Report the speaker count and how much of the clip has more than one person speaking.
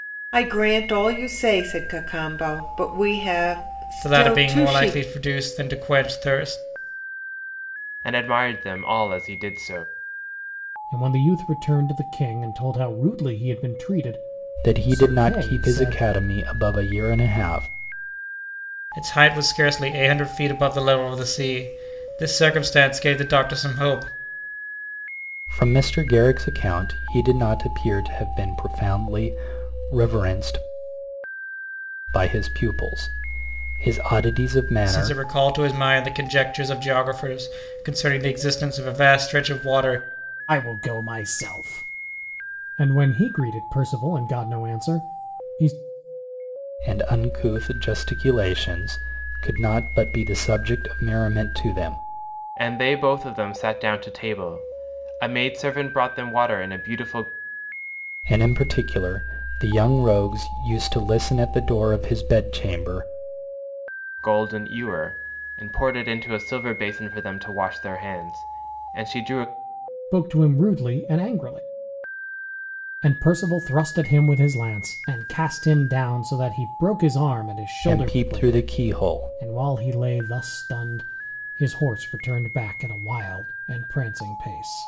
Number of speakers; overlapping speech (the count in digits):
5, about 5%